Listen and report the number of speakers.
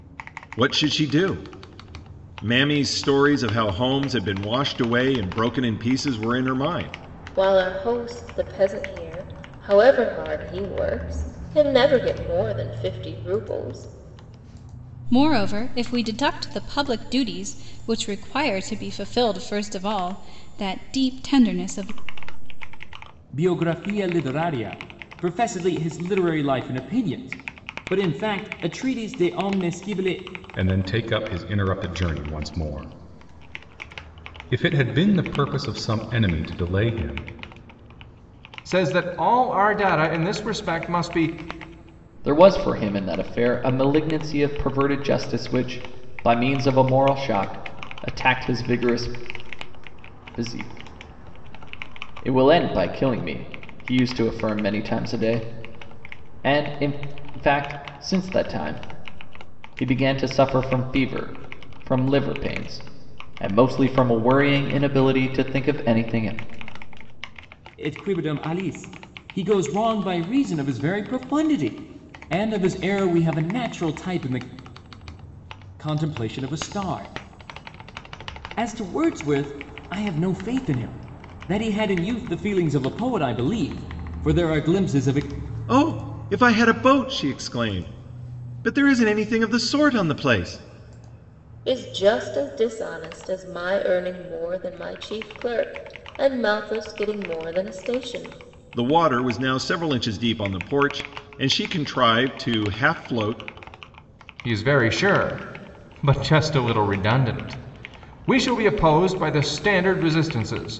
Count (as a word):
seven